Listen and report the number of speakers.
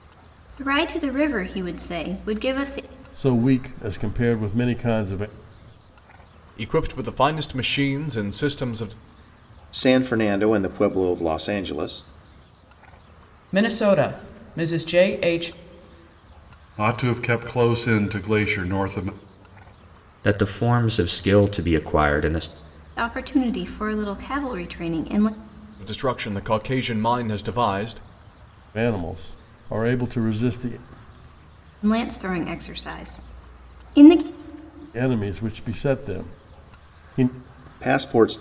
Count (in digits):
7